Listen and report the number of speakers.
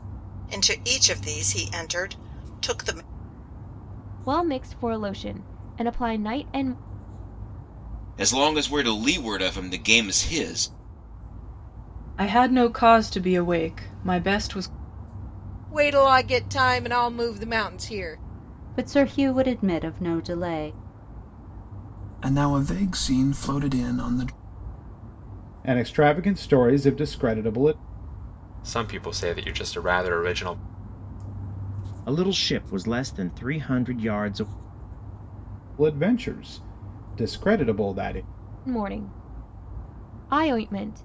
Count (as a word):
ten